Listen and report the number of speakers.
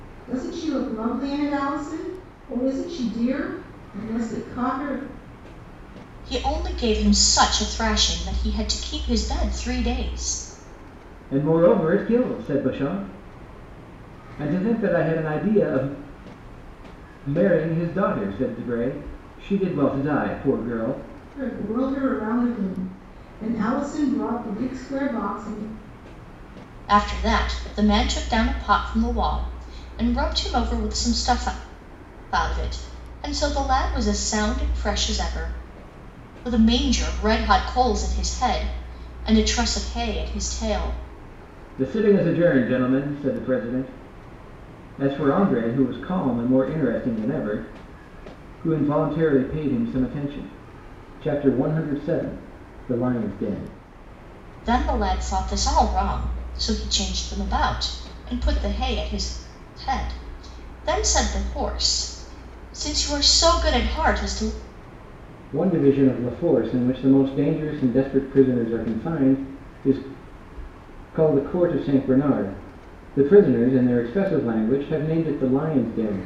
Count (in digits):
3